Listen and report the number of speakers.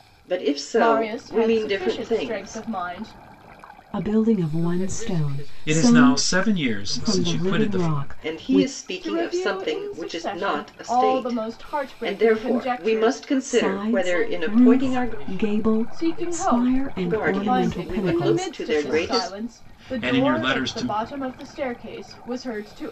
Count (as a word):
five